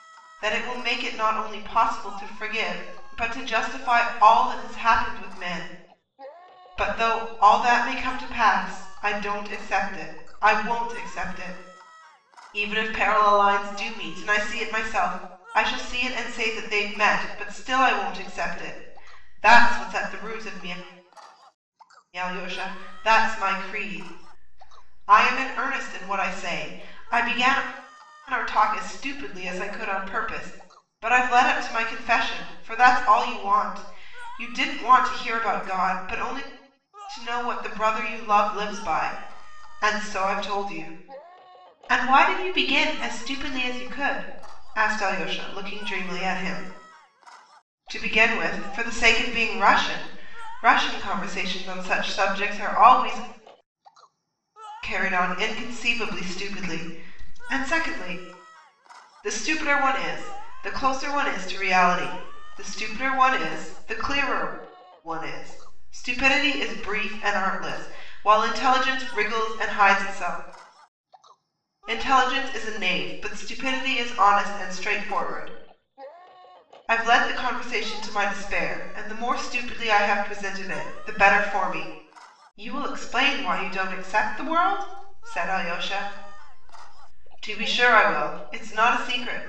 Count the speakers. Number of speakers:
1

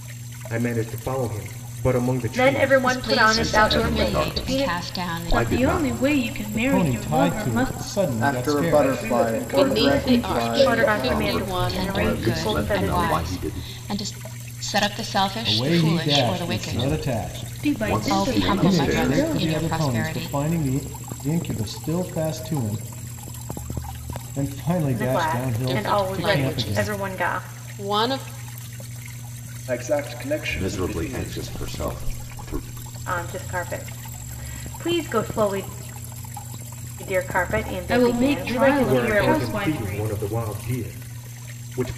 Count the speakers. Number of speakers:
9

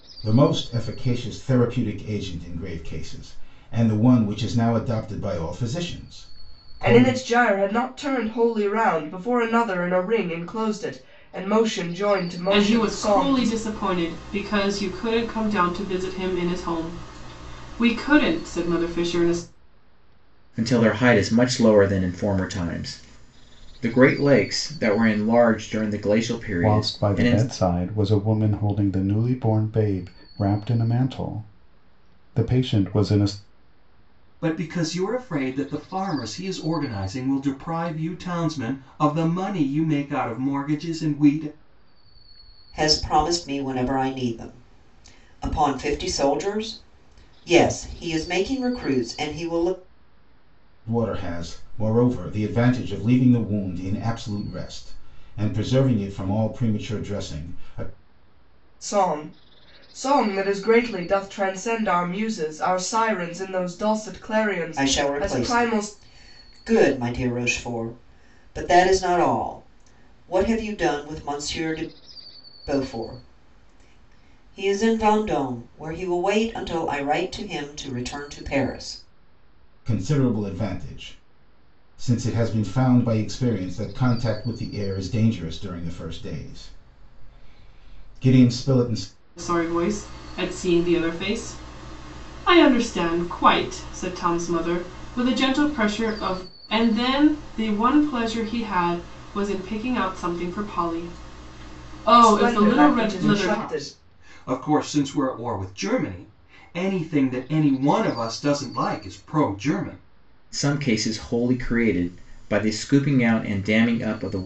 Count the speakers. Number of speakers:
7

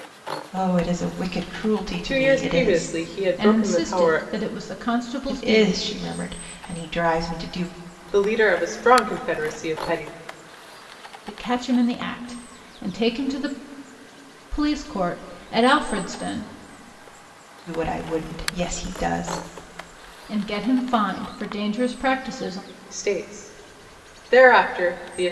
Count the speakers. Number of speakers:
3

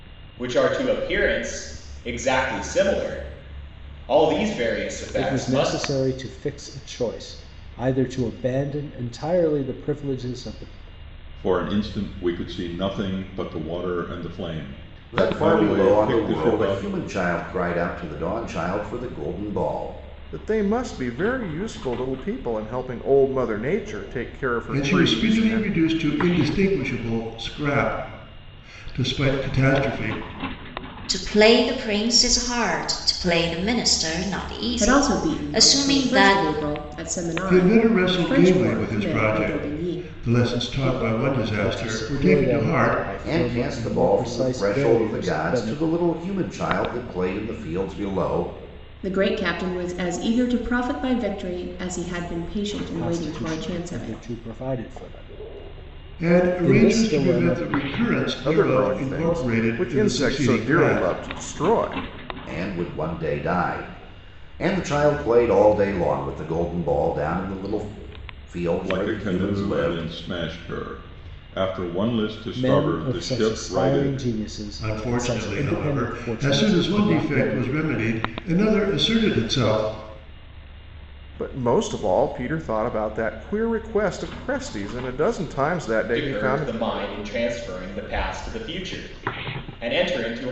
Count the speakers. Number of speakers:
8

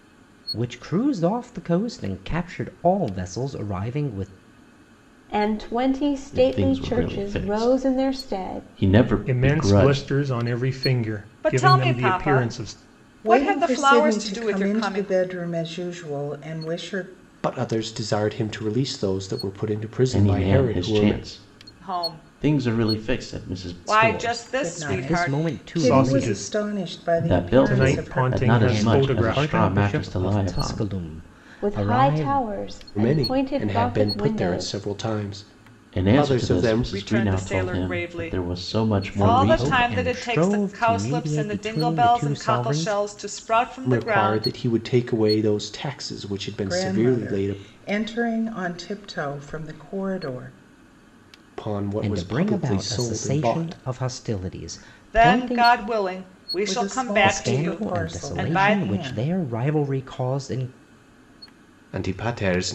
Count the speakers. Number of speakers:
7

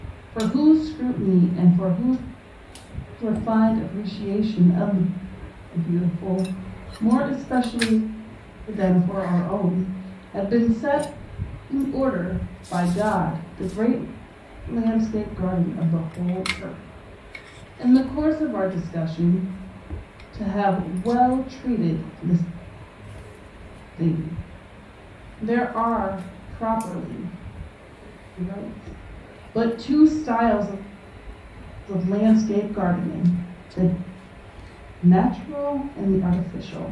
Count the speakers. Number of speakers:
1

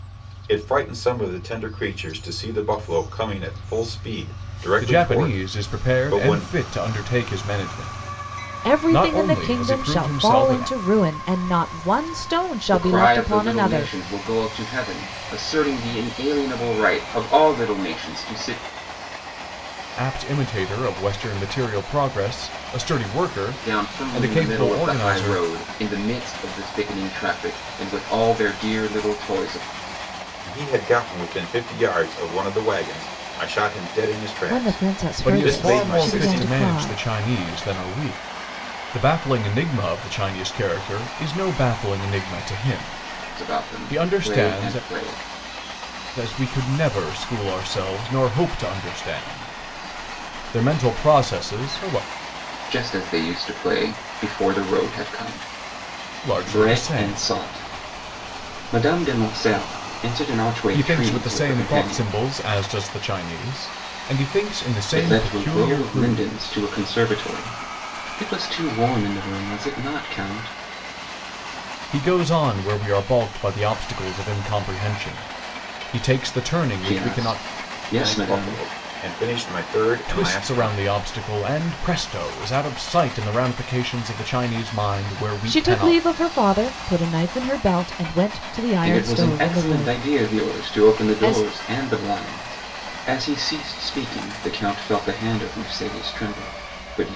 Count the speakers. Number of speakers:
4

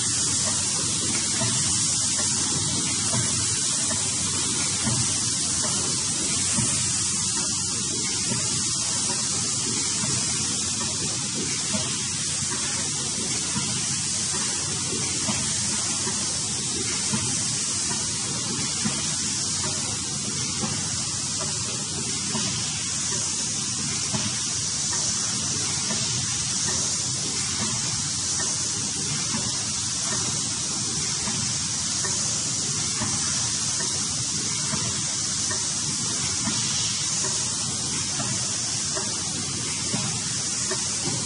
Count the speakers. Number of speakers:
0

